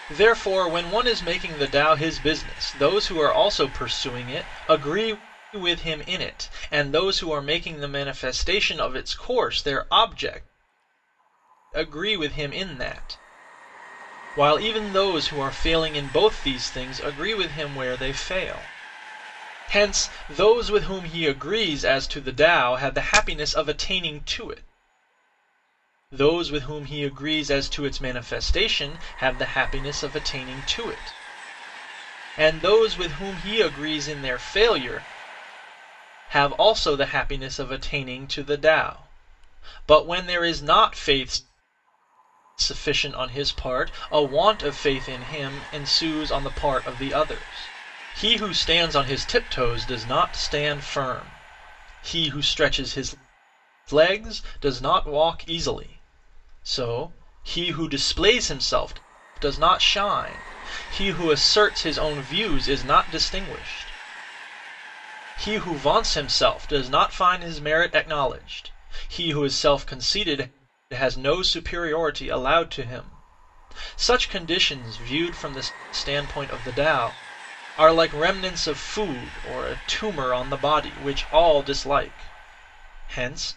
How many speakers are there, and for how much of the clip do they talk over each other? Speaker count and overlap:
1, no overlap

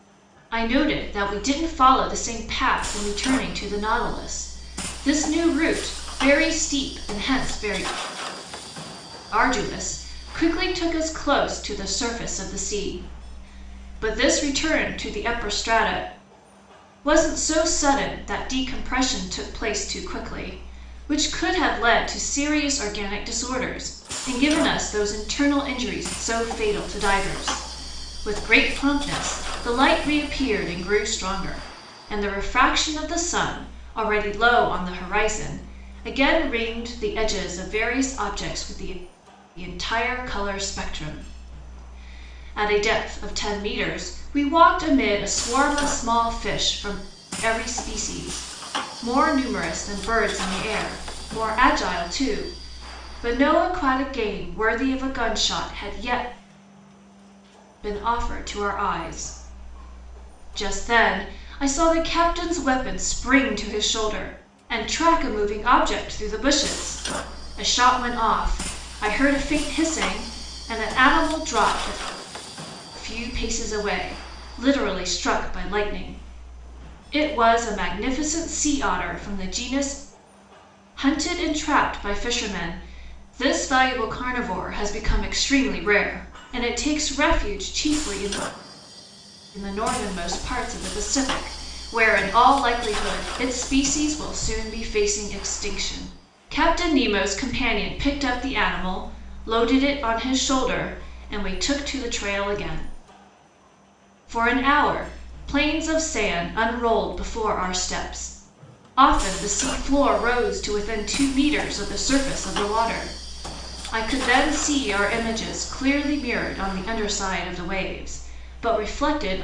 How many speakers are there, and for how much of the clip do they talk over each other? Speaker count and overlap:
1, no overlap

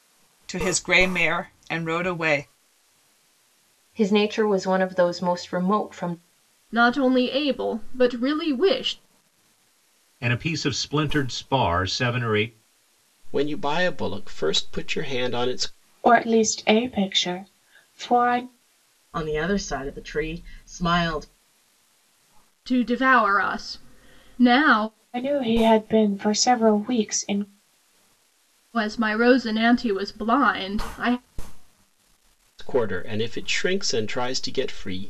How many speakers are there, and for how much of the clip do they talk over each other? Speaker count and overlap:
7, no overlap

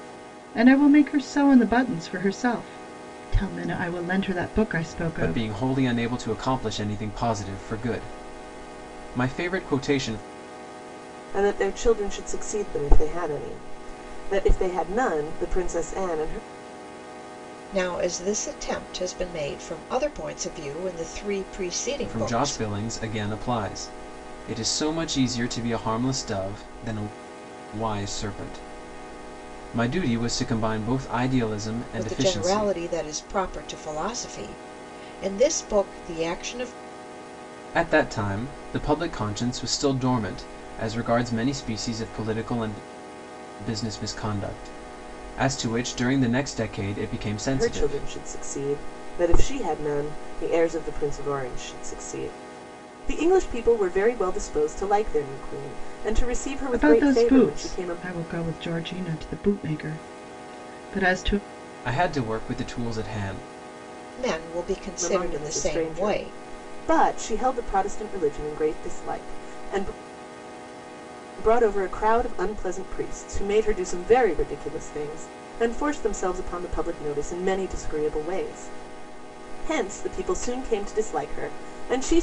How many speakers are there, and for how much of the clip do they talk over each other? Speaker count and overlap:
4, about 6%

